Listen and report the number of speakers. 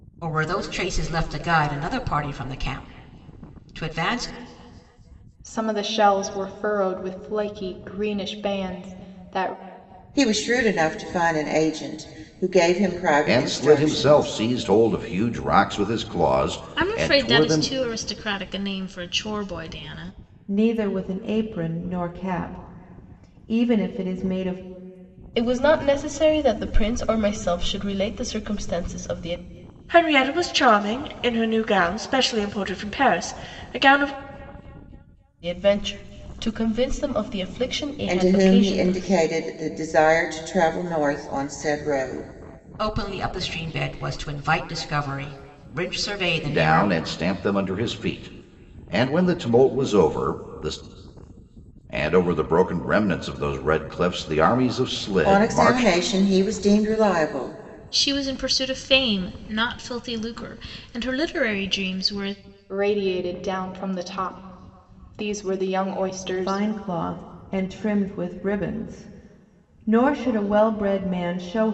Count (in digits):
8